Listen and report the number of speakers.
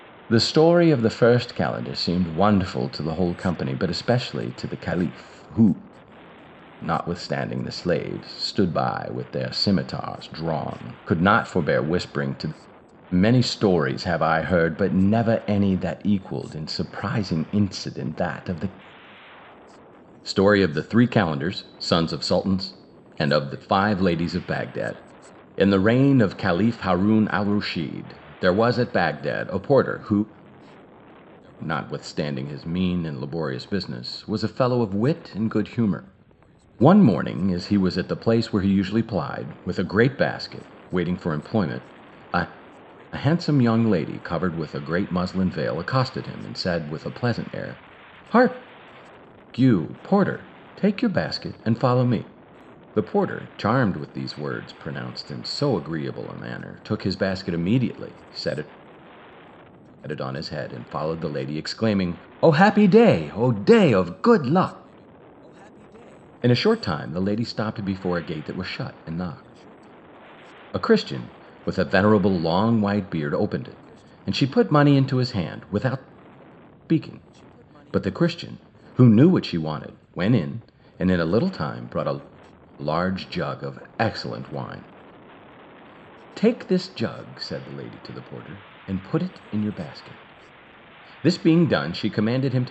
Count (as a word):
one